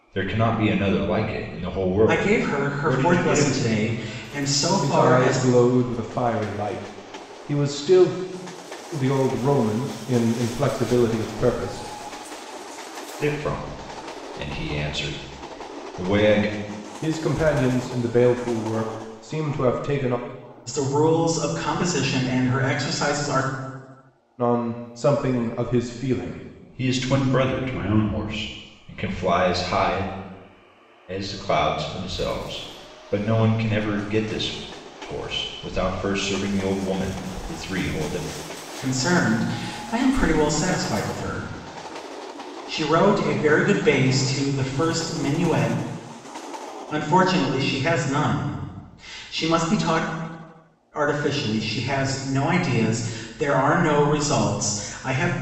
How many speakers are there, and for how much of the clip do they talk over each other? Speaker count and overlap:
three, about 4%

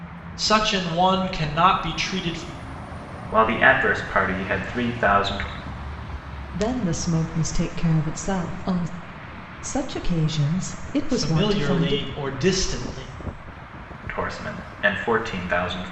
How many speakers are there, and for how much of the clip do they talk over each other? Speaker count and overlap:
three, about 6%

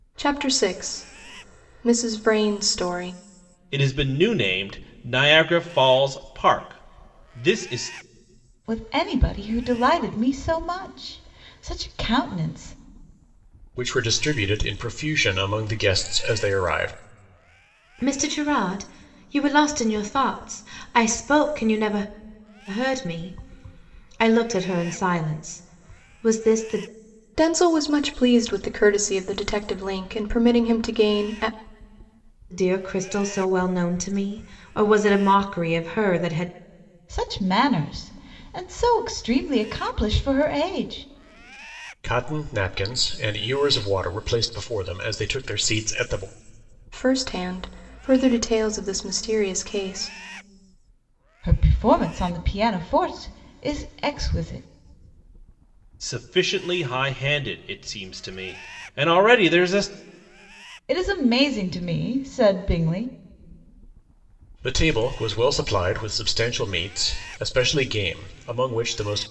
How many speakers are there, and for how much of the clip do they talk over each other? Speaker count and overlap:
five, no overlap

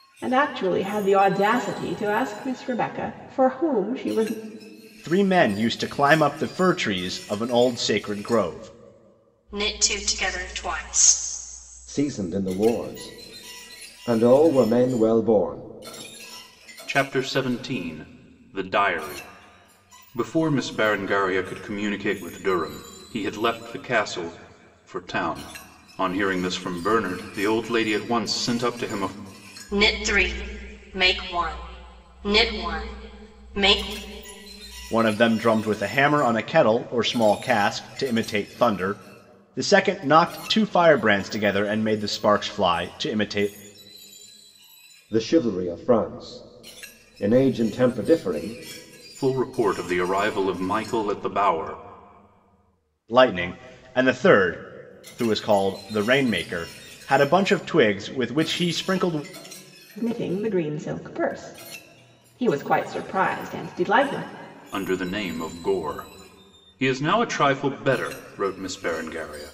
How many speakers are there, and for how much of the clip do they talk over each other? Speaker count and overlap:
five, no overlap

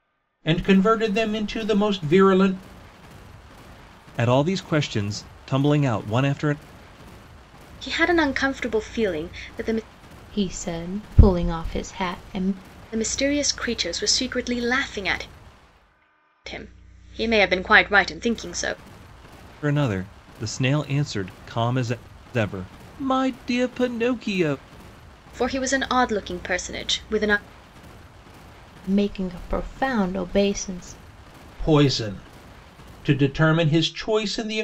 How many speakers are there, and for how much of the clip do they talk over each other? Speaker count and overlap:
four, no overlap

